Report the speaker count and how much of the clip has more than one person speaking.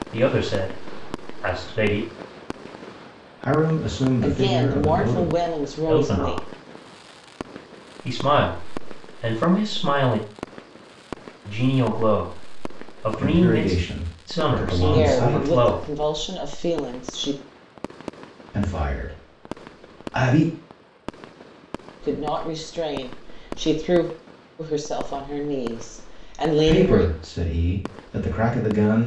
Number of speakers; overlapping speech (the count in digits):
3, about 15%